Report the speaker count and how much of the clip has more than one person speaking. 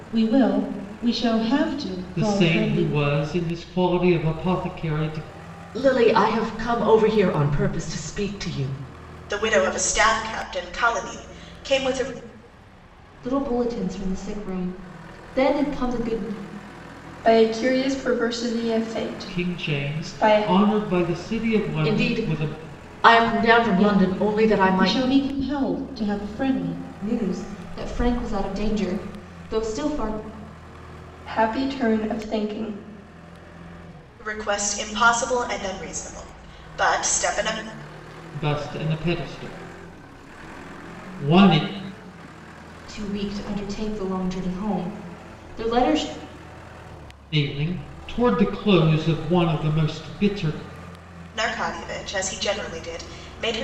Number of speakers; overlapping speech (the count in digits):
6, about 8%